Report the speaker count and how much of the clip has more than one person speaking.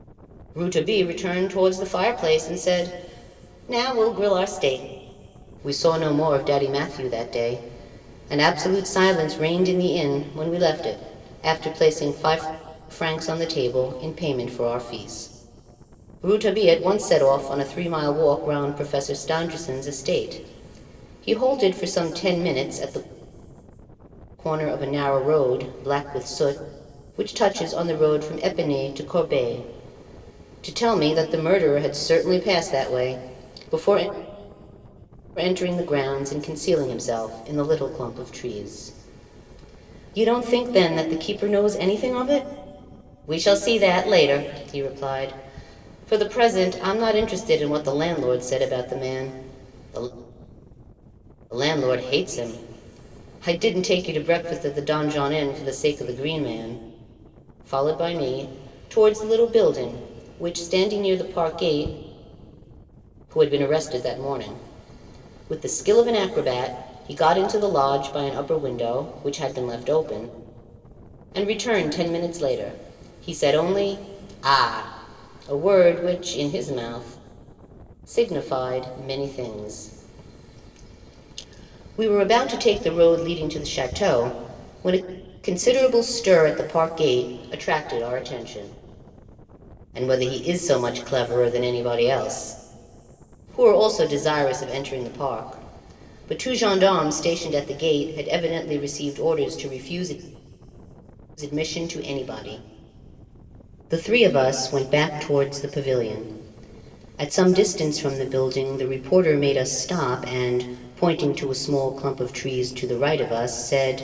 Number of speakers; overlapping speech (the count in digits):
1, no overlap